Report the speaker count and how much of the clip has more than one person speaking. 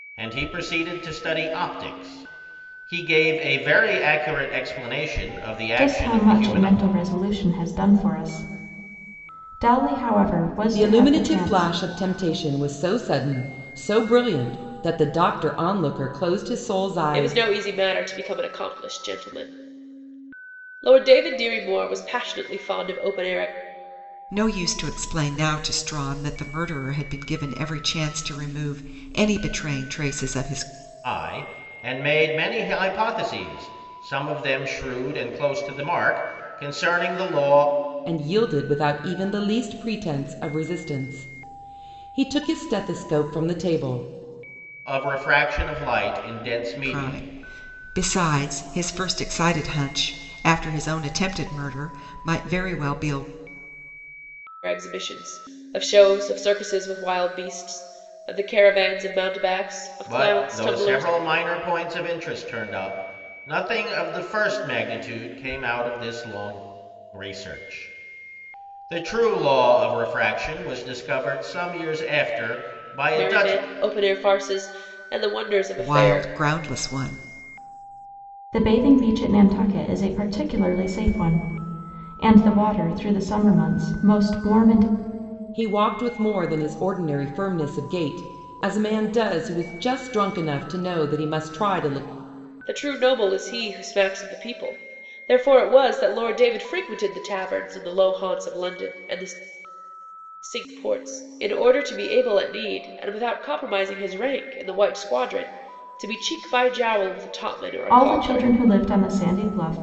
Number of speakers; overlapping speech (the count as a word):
five, about 5%